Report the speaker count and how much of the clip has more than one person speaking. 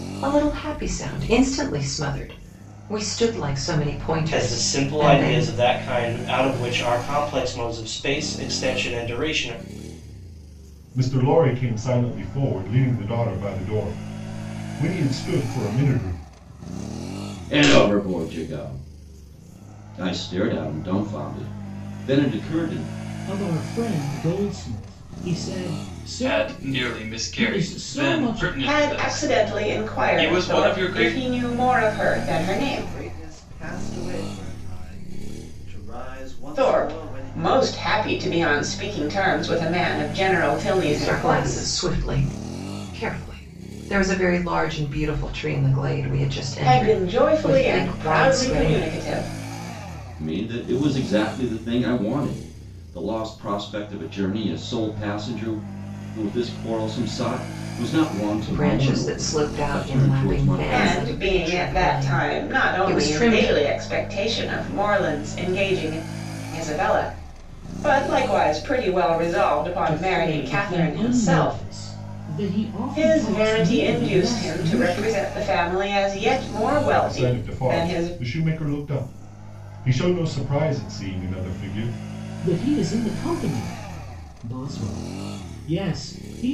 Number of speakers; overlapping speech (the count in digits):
8, about 25%